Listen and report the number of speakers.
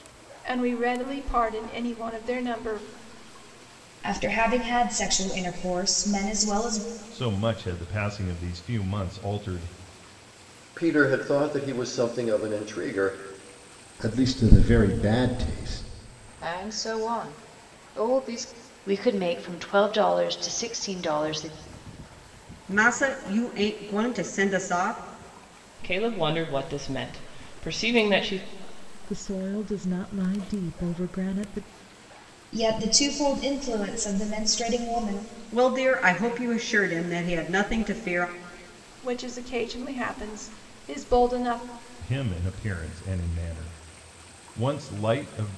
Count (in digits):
10